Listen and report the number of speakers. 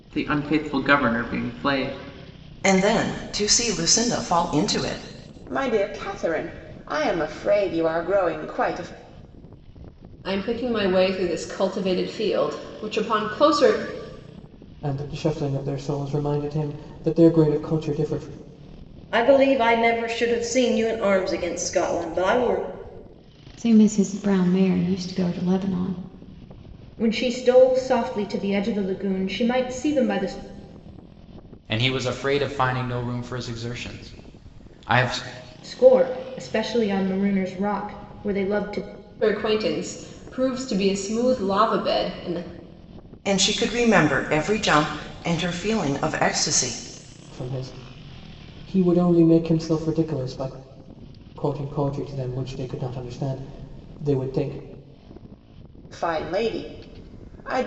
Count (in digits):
9